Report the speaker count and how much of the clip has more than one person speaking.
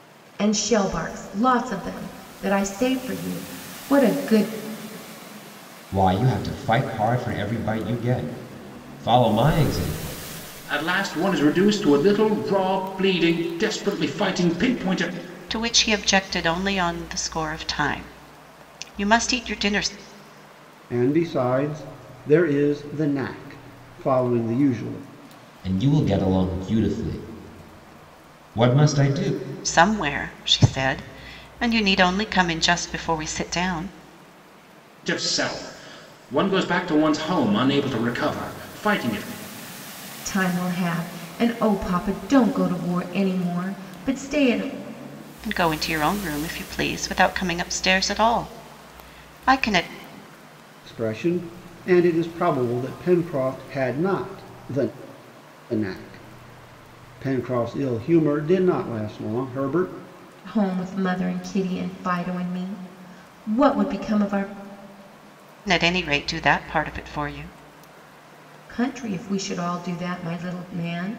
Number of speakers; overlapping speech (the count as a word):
five, no overlap